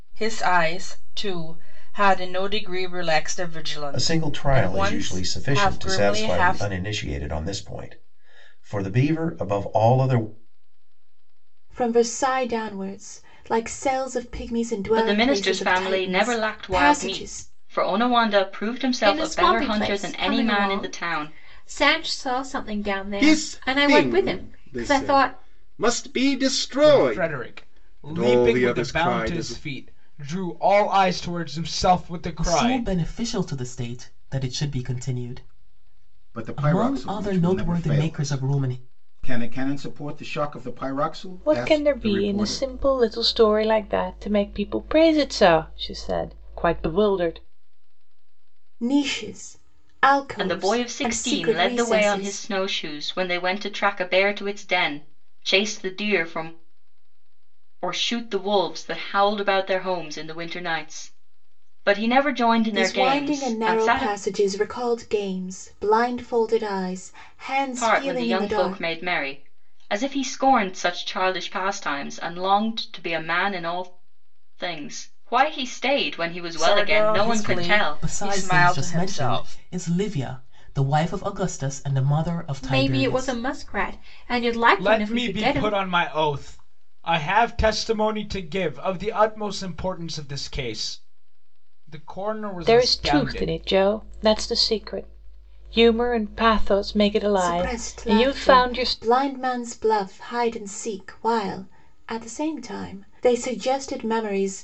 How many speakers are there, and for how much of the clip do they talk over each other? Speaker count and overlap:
ten, about 28%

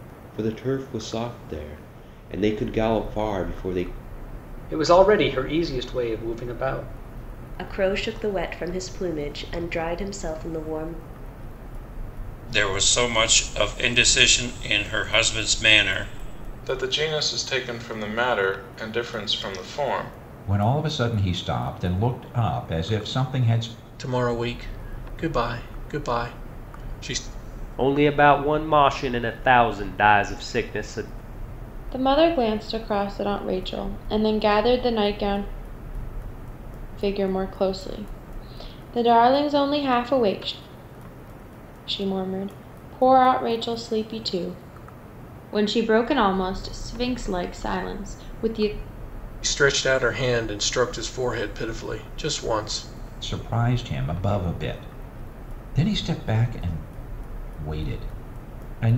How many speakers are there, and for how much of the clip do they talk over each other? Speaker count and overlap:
nine, no overlap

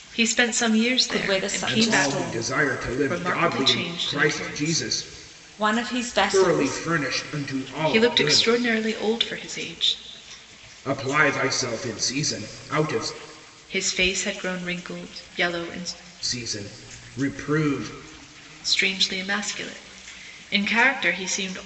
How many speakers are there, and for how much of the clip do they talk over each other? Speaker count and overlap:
three, about 21%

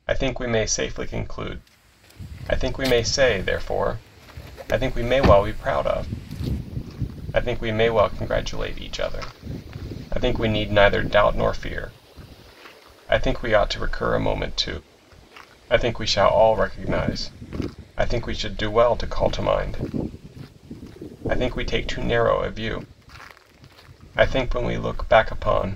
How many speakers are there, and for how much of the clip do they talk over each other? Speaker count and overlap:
one, no overlap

